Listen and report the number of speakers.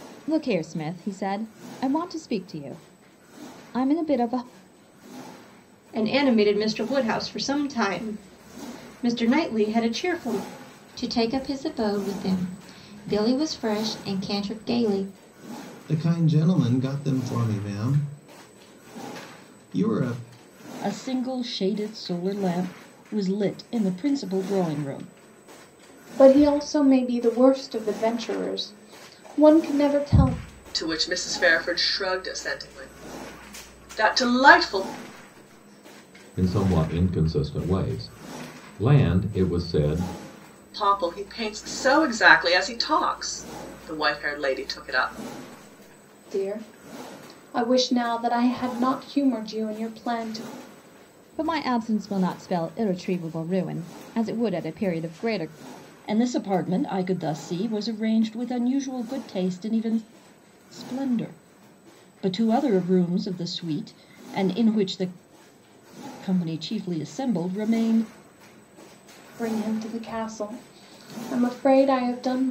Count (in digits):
8